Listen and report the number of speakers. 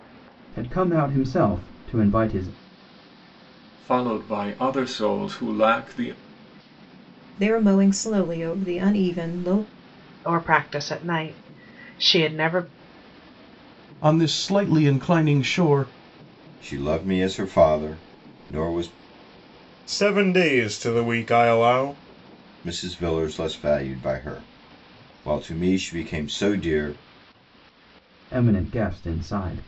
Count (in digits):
7